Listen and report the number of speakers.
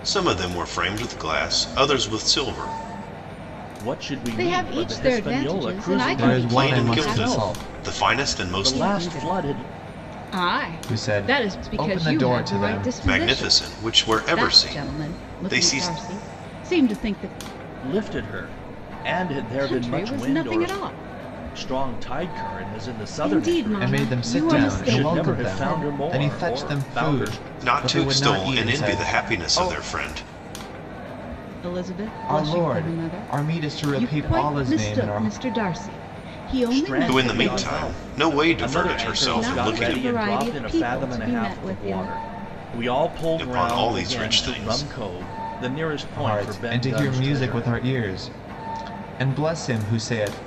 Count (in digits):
4